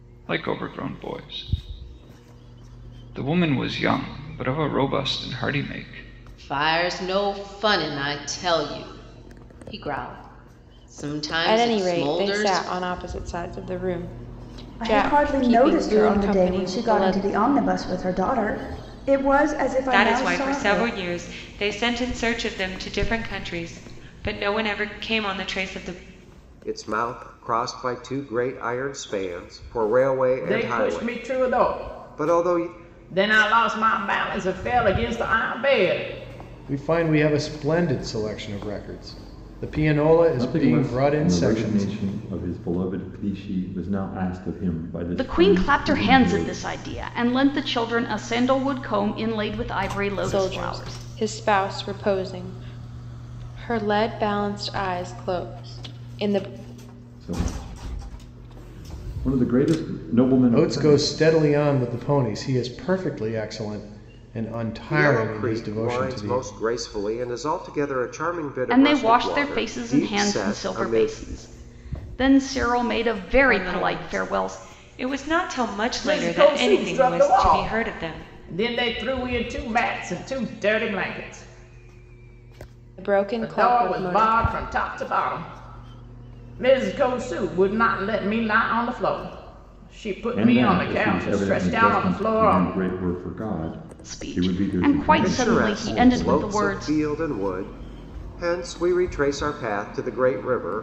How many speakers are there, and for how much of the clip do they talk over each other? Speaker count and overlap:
10, about 26%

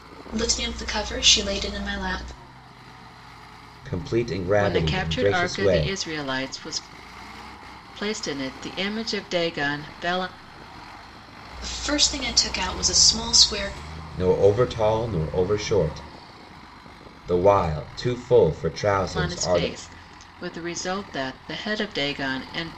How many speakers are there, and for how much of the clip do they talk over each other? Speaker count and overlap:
3, about 9%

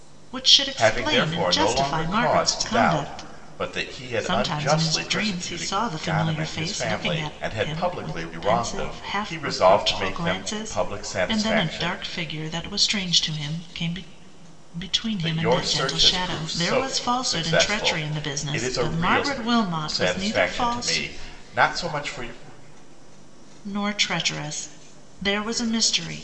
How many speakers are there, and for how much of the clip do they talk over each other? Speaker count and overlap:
2, about 59%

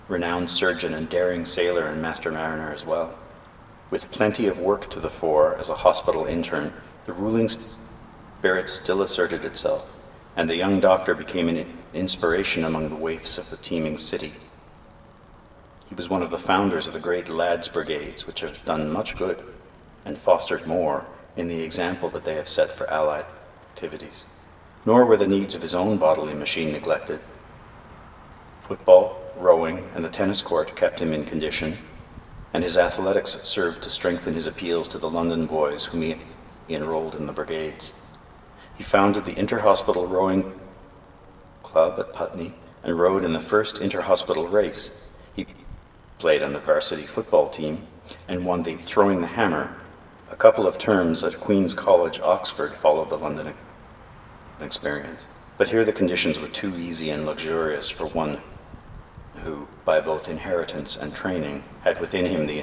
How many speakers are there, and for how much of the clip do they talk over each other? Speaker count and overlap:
1, no overlap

